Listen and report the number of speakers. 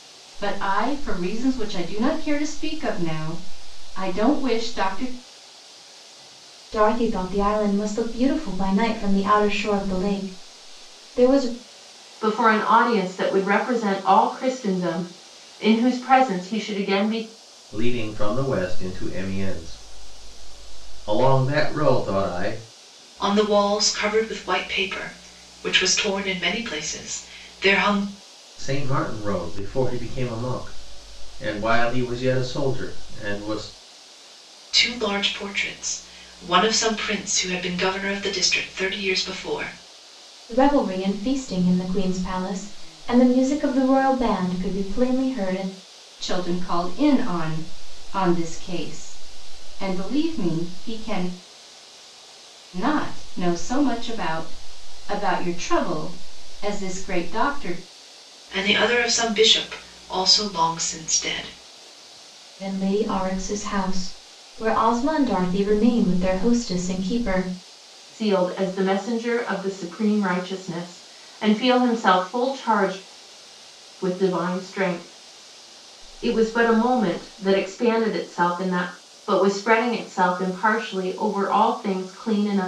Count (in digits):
5